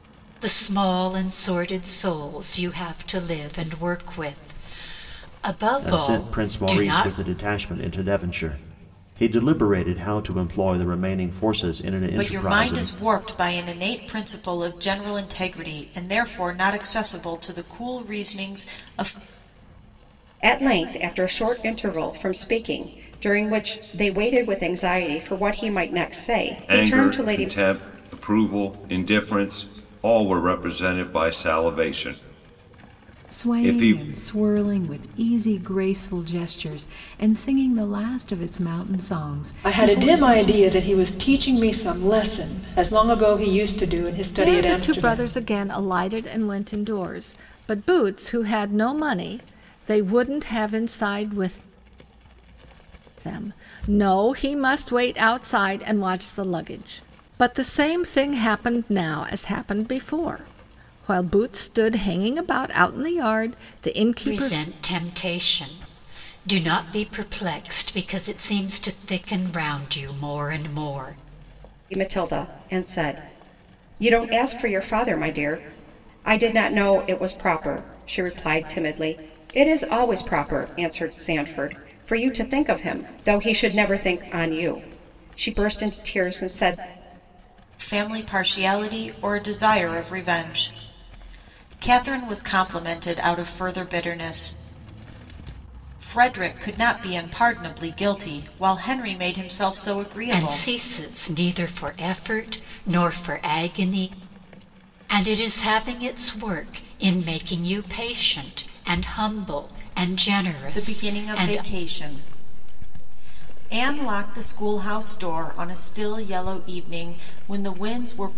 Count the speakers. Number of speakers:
8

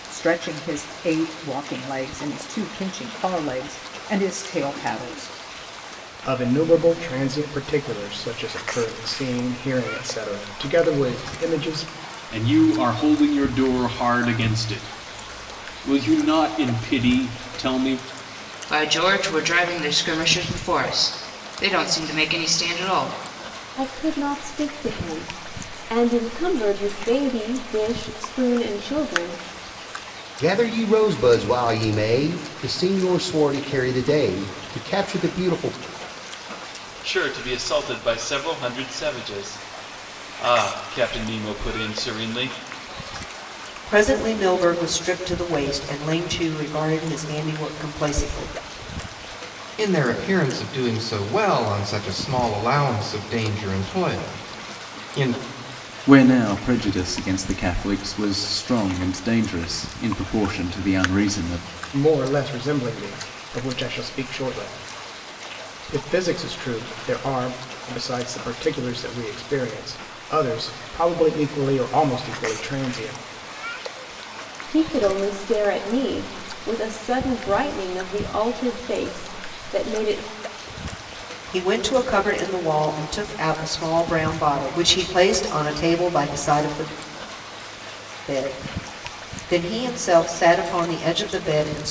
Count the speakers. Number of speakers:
10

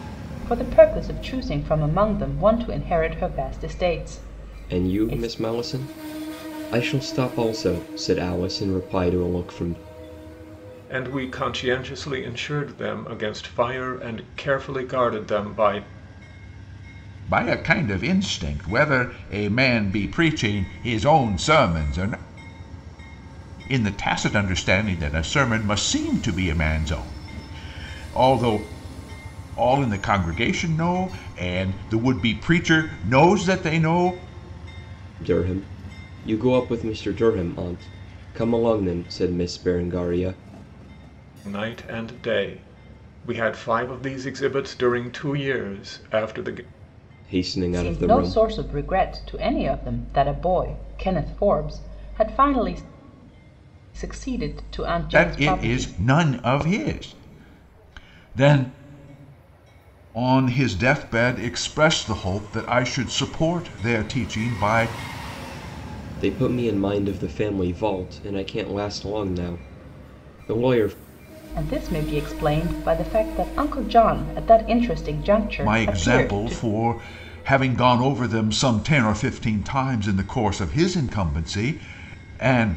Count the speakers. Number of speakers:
4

